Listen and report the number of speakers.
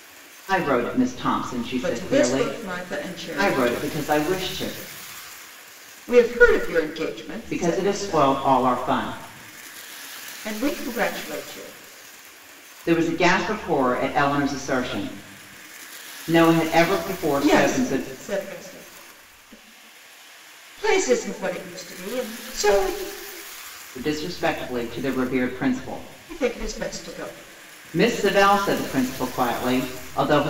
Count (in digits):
2